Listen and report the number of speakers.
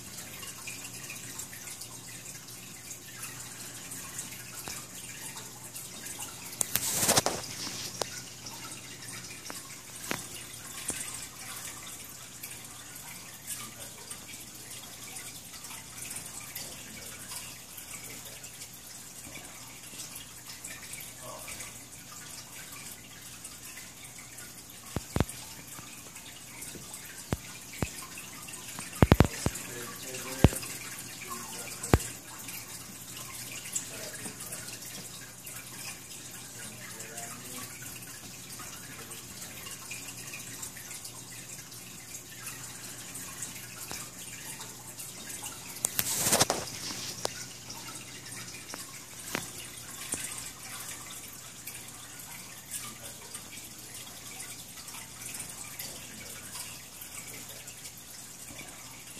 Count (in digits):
0